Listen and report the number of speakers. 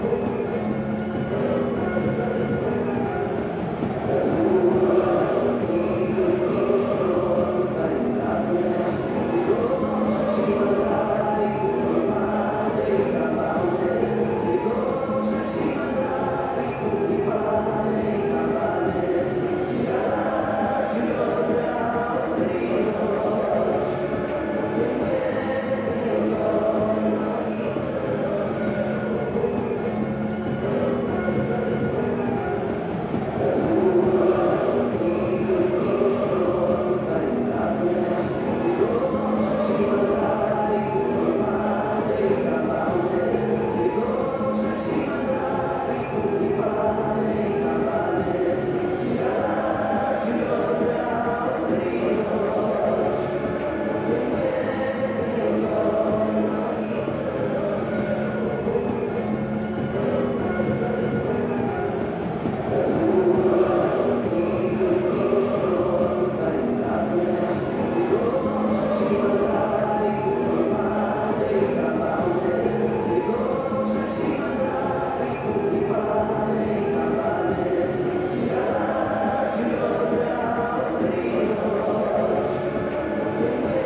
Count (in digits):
0